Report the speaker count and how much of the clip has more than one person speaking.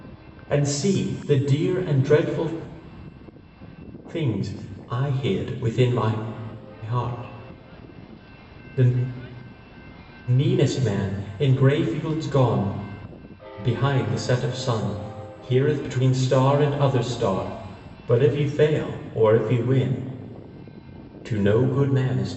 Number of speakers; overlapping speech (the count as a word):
one, no overlap